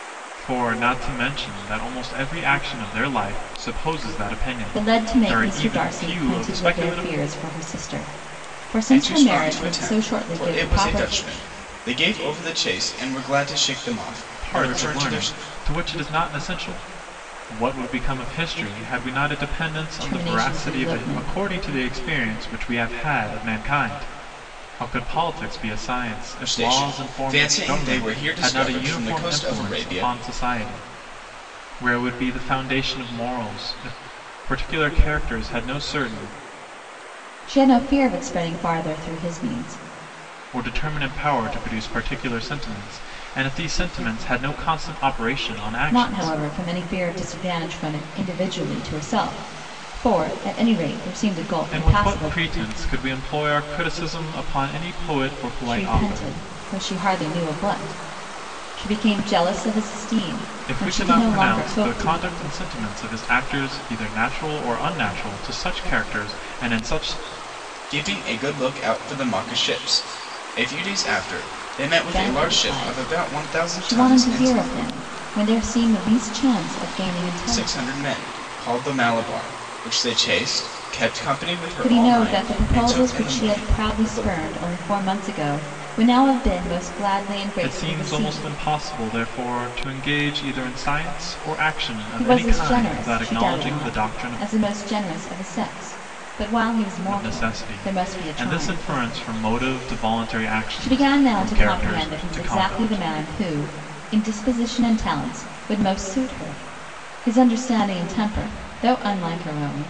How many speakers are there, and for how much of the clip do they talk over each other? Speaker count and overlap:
3, about 25%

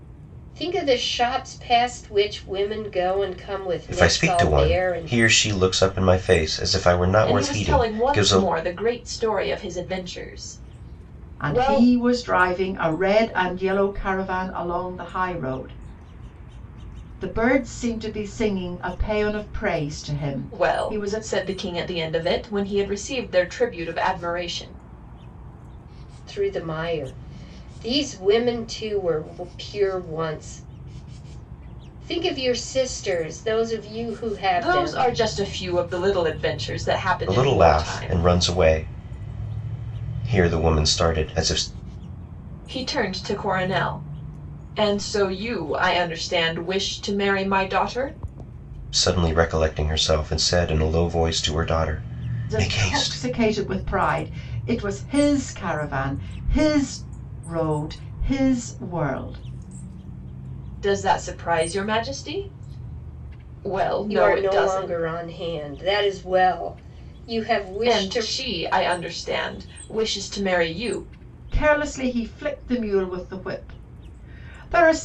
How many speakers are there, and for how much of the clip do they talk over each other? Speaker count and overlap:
4, about 10%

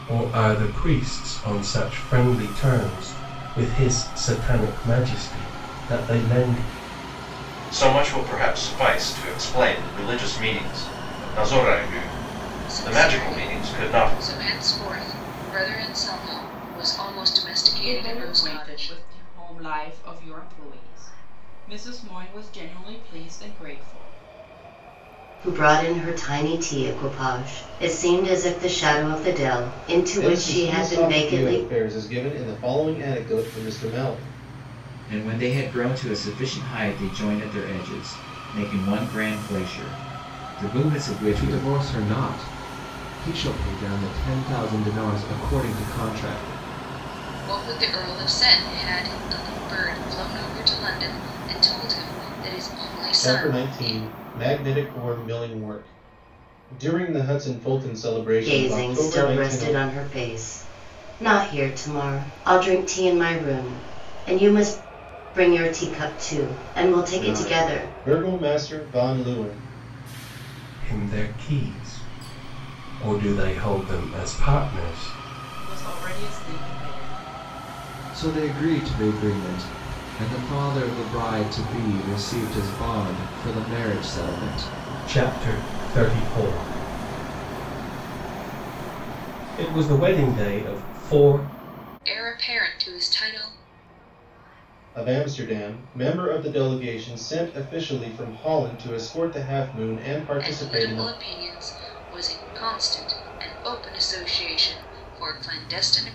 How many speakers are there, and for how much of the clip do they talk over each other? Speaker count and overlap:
8, about 8%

